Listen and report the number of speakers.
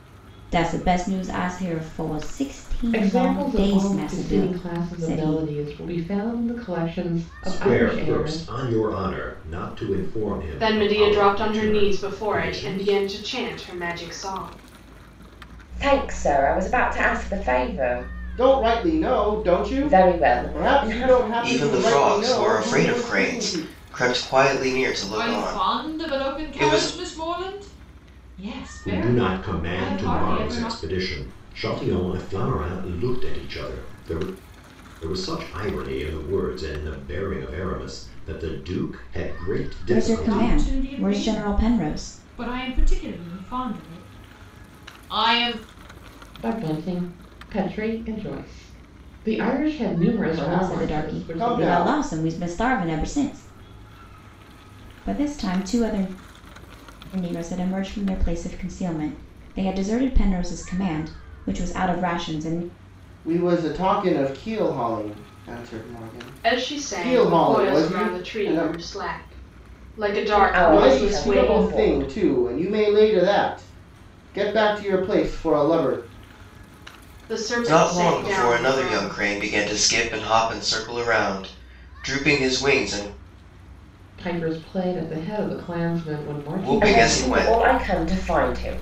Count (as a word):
eight